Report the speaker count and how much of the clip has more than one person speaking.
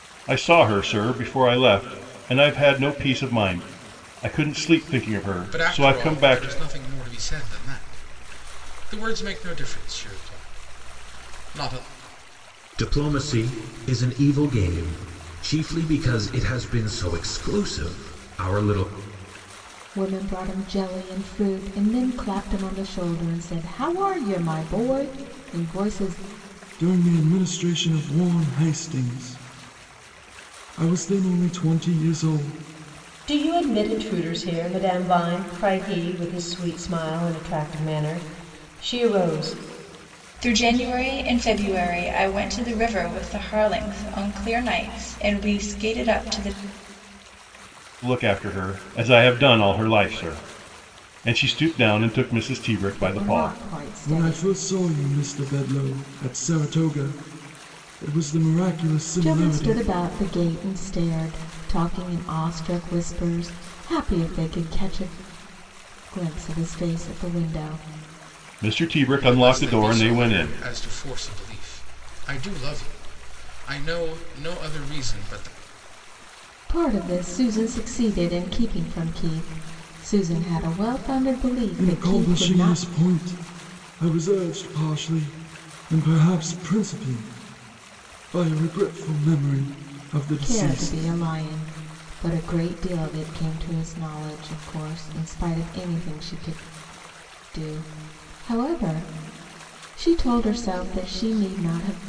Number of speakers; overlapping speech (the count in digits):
7, about 6%